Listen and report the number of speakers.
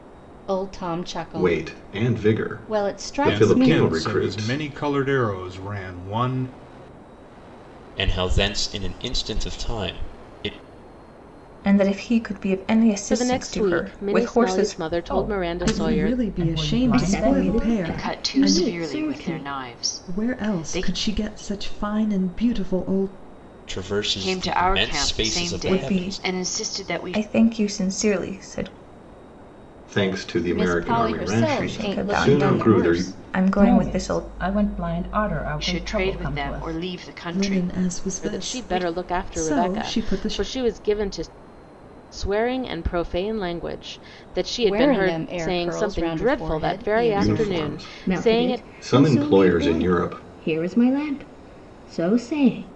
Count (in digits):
10